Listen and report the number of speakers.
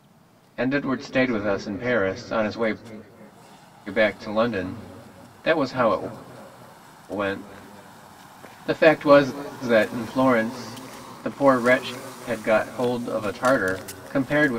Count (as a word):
one